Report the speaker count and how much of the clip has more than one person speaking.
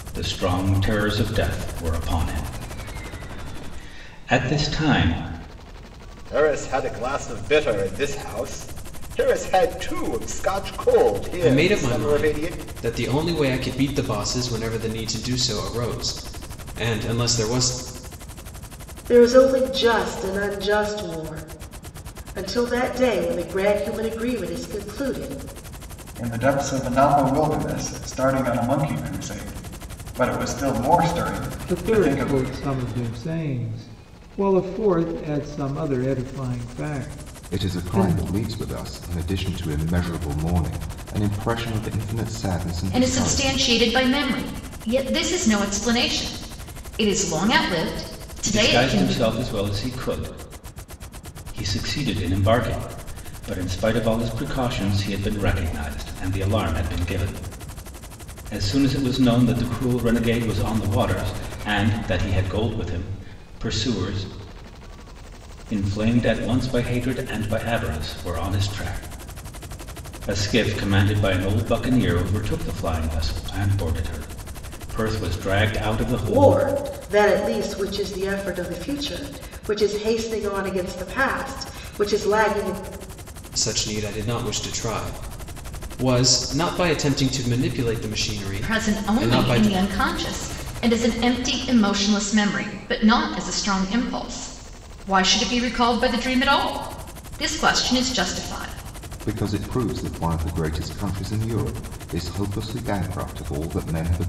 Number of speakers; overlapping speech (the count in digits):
8, about 6%